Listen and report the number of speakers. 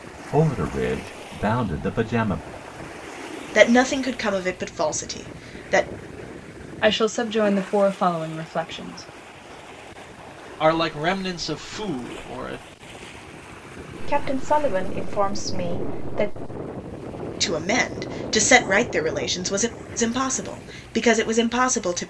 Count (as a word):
five